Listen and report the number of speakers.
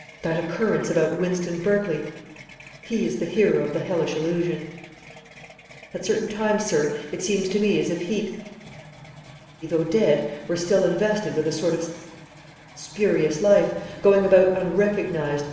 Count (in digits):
1